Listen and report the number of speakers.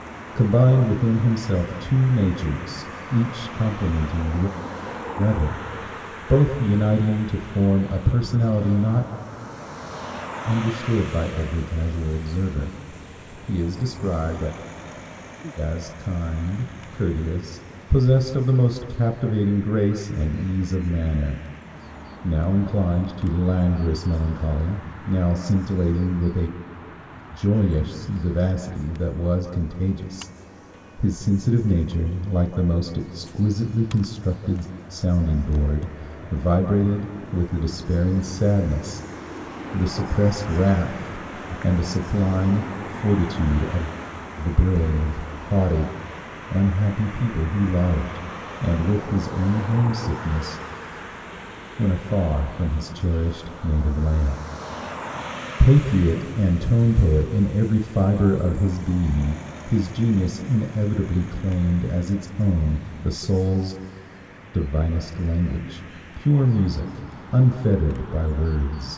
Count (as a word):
one